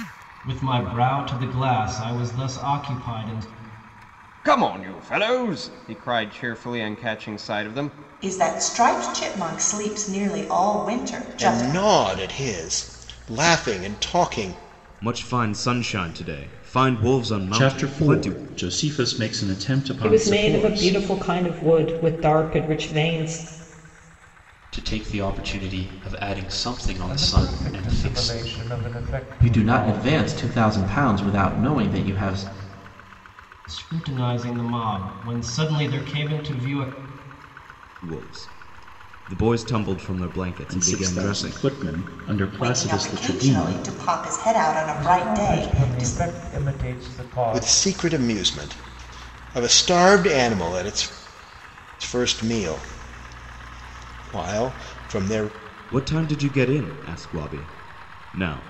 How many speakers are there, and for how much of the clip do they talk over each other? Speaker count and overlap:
10, about 14%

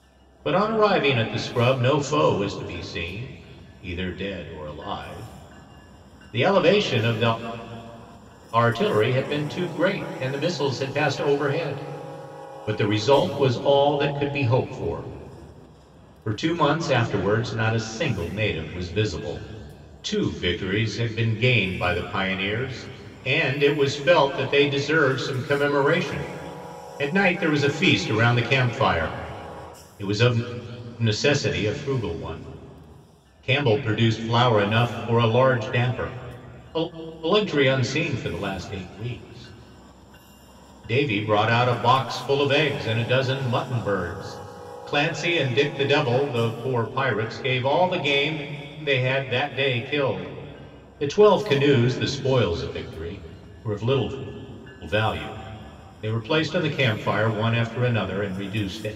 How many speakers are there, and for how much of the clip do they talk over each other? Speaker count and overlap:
1, no overlap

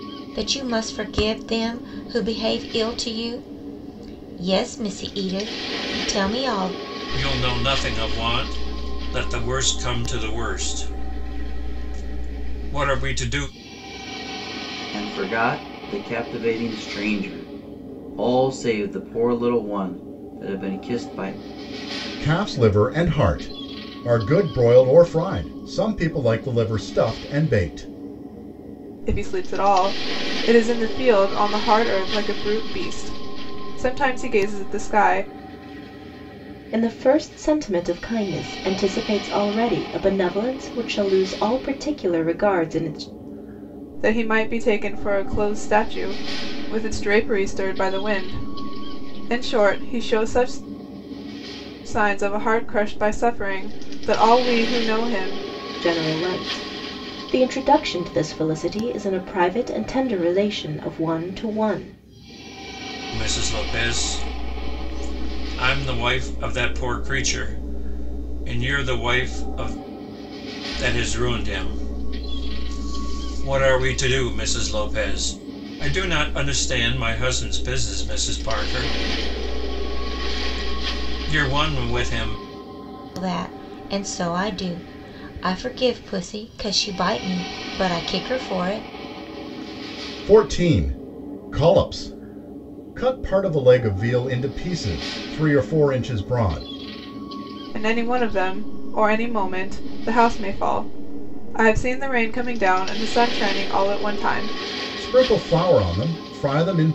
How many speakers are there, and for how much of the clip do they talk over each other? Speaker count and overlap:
6, no overlap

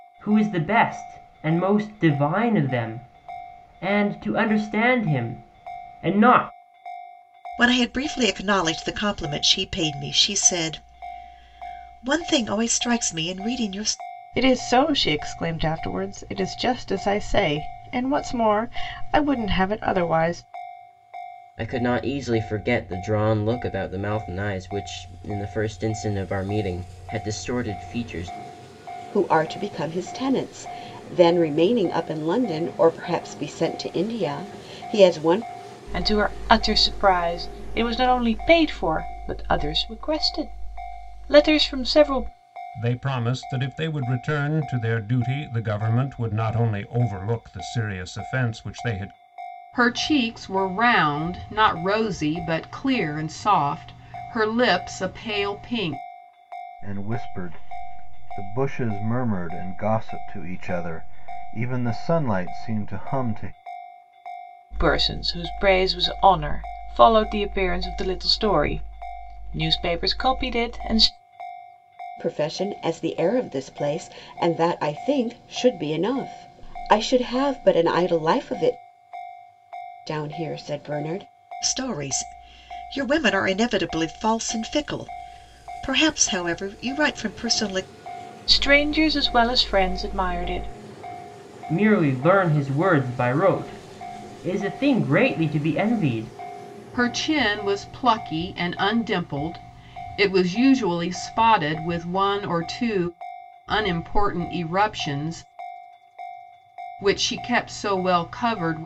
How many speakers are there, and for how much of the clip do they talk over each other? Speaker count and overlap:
9, no overlap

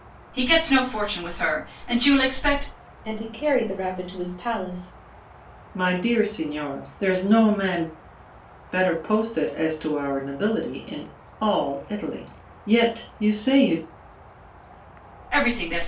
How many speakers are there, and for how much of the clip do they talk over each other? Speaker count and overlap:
3, no overlap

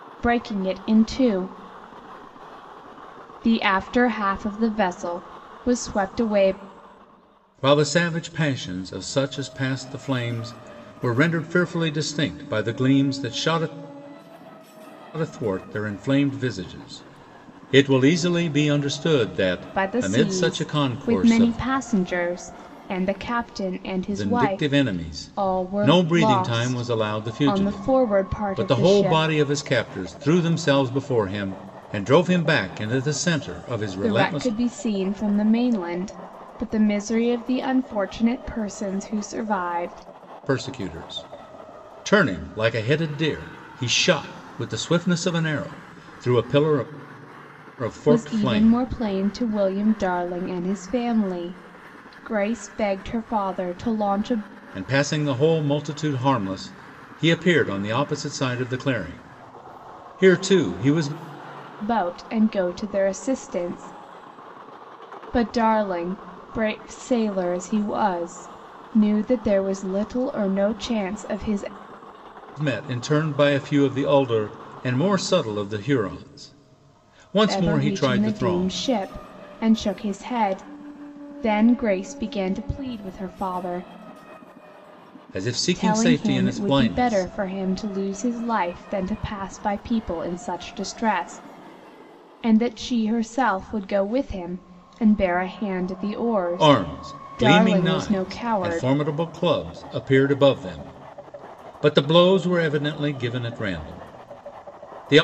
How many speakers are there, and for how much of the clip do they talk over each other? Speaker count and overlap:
2, about 13%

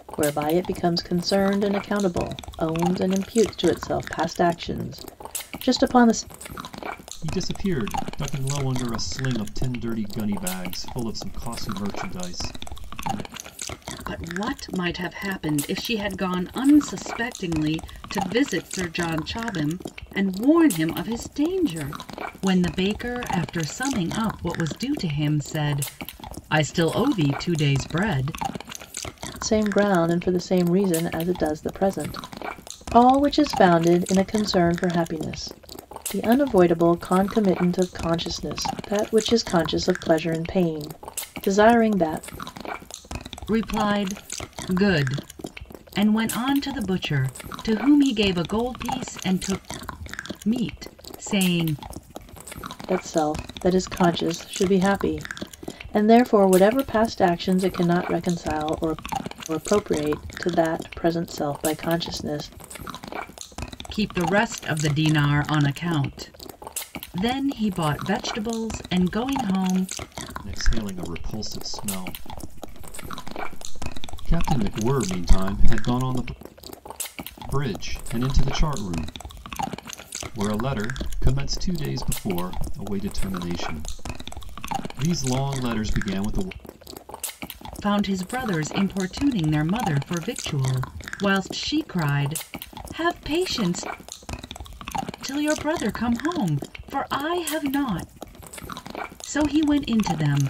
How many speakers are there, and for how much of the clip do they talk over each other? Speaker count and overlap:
3, no overlap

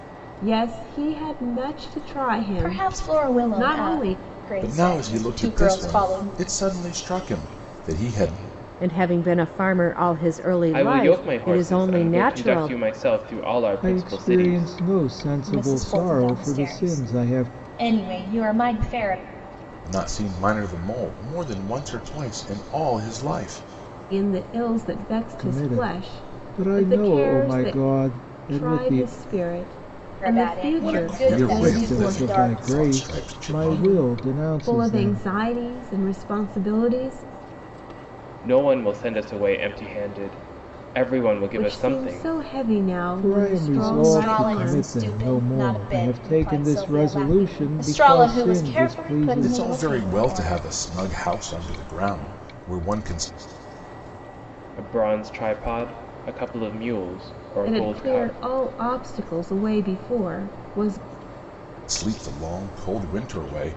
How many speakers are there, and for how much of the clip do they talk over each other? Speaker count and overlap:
6, about 41%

